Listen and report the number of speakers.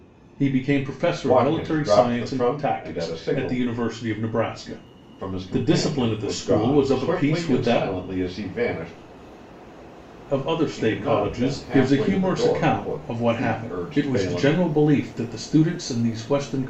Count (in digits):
2